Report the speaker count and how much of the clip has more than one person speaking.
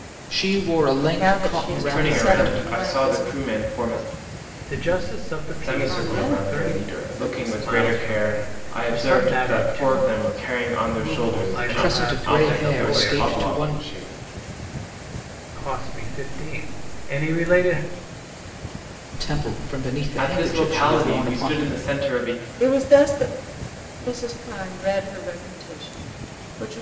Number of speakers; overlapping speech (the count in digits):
4, about 44%